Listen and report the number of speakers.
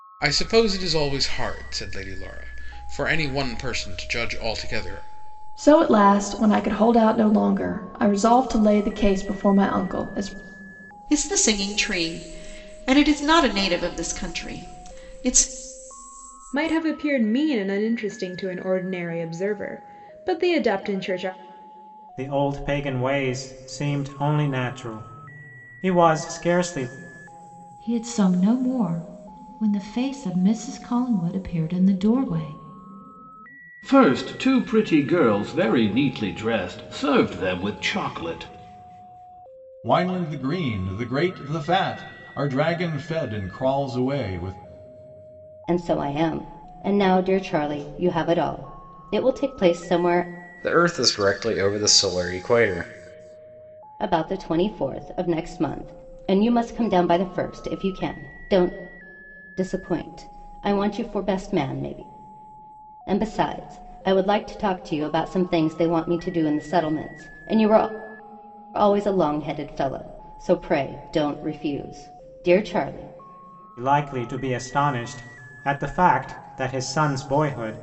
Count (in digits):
10